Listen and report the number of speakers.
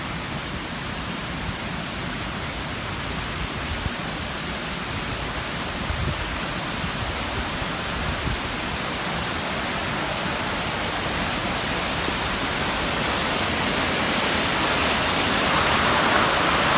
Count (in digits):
0